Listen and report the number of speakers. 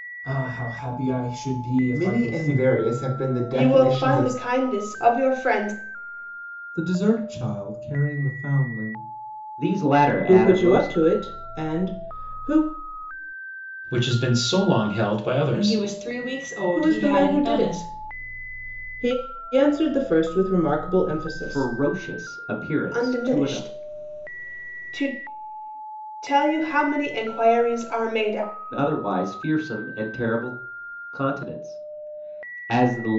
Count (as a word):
eight